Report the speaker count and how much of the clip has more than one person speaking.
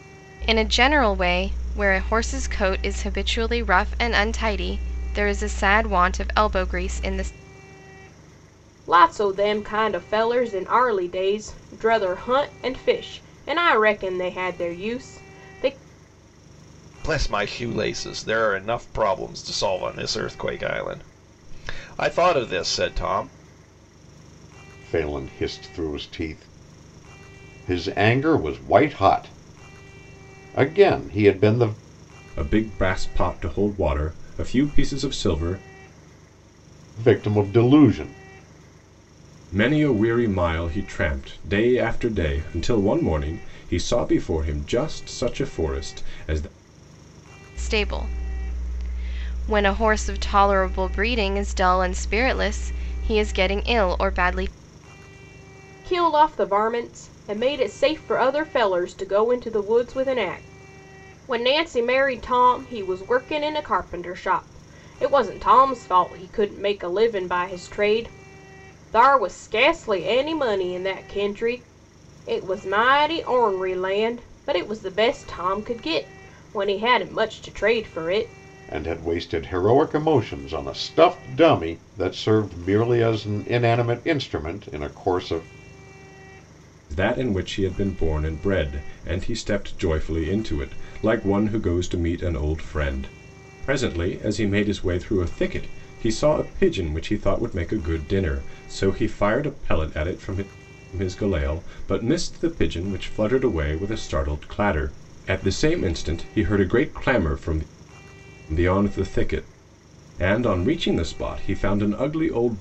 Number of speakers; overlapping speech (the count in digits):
5, no overlap